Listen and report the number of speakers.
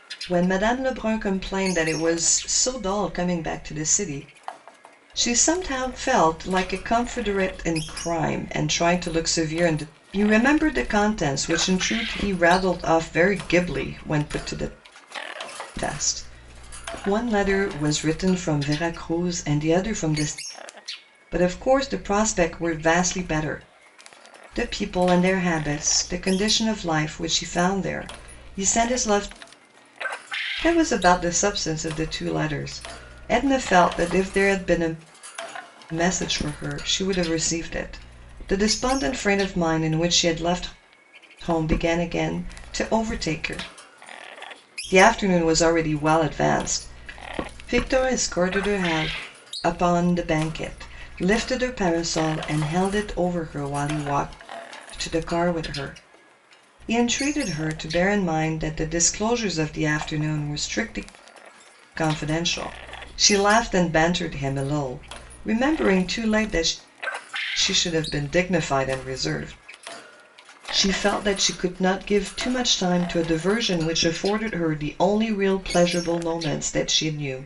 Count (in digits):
1